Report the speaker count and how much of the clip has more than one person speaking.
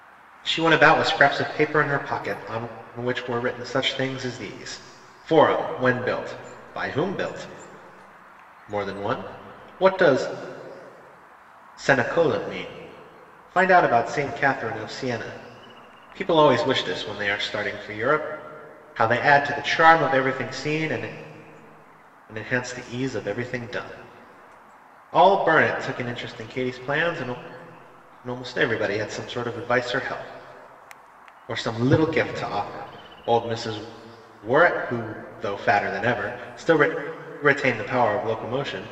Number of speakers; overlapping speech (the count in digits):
1, no overlap